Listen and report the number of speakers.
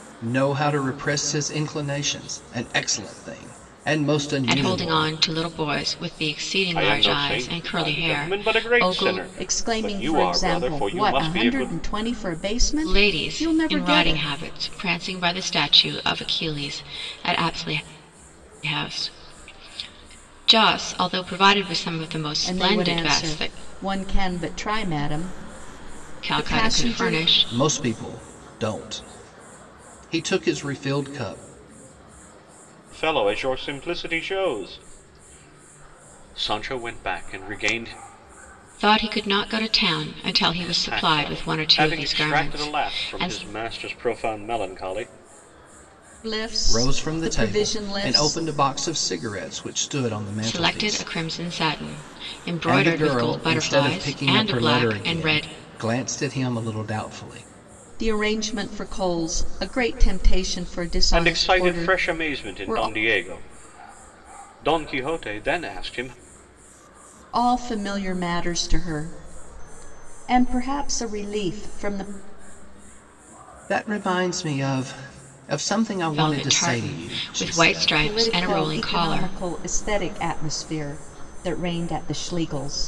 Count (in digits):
4